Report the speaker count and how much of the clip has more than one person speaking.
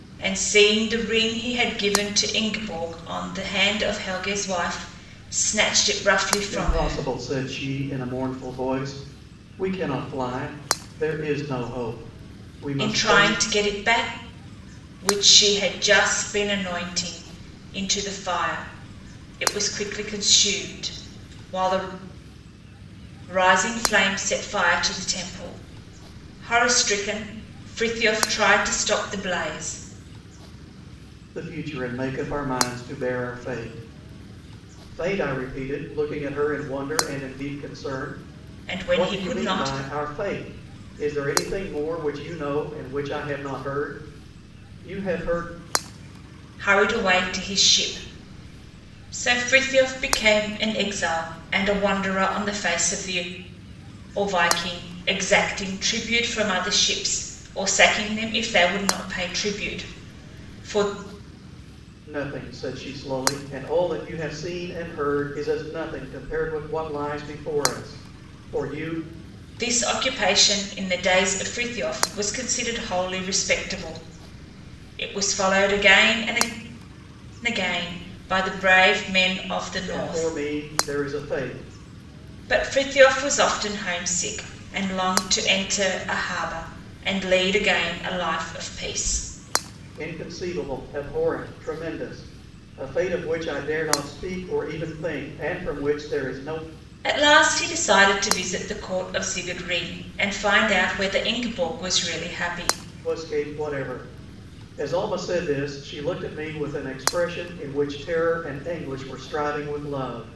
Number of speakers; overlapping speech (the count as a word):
two, about 2%